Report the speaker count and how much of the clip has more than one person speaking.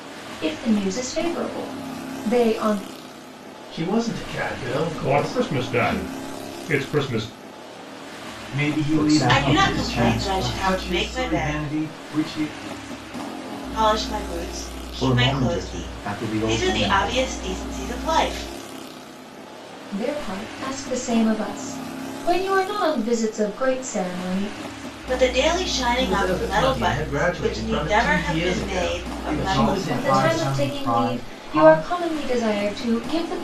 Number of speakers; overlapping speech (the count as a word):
six, about 35%